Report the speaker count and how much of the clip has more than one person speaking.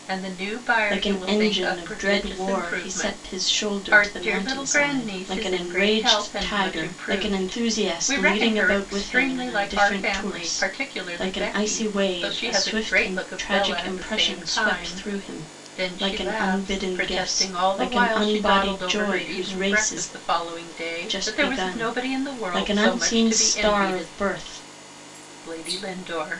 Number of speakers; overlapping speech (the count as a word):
two, about 78%